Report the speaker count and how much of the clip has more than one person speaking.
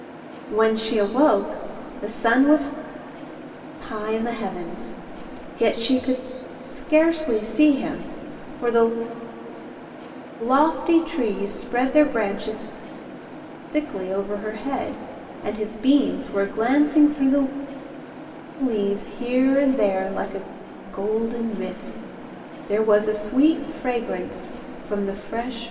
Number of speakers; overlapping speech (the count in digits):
1, no overlap